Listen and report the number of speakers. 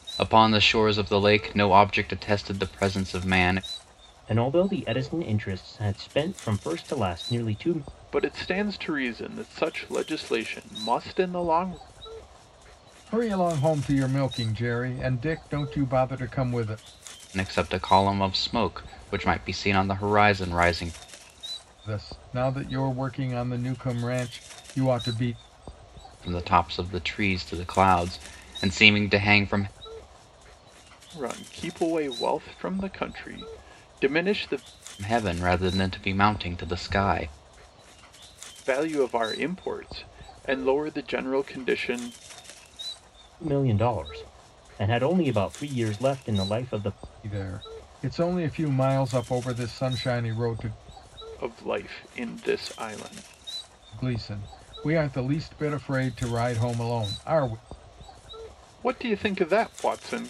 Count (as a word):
four